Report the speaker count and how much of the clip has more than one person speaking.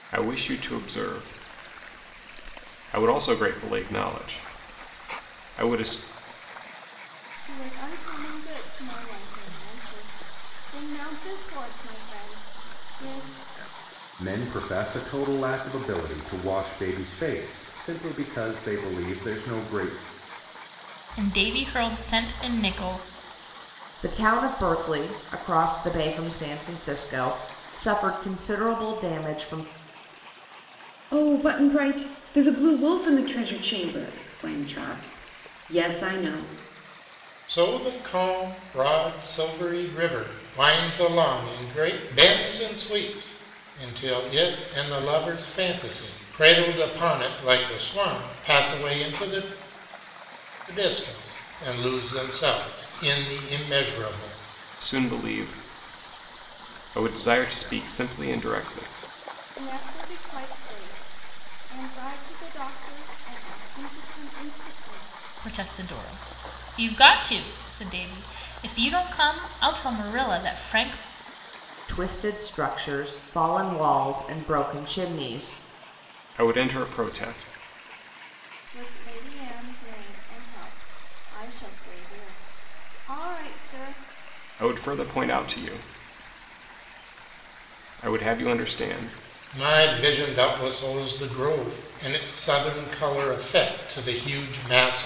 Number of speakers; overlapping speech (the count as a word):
seven, no overlap